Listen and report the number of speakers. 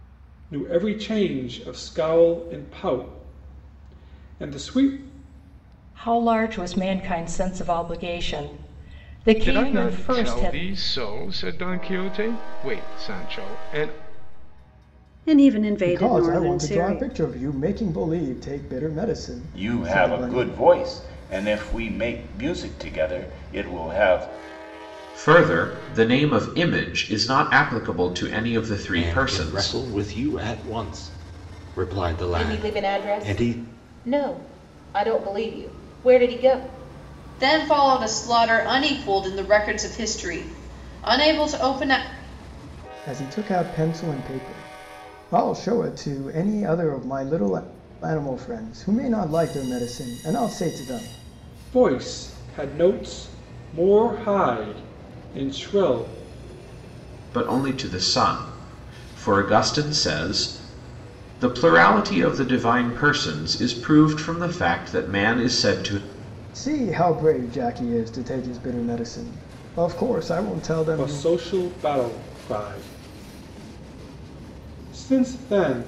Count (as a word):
ten